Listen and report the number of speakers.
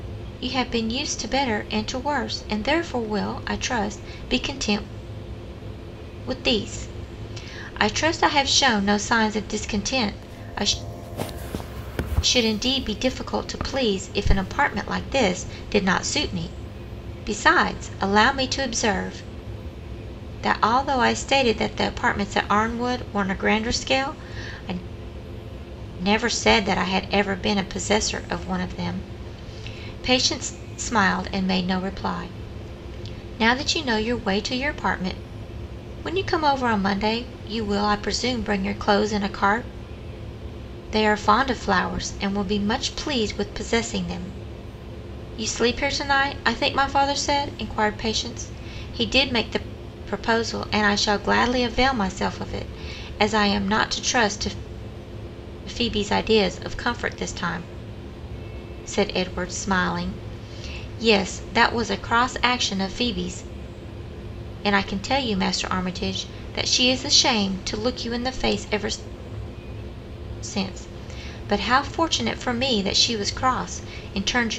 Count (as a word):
one